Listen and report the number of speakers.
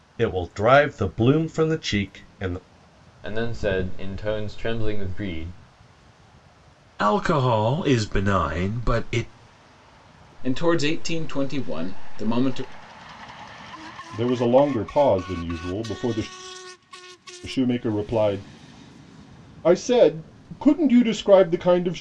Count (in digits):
5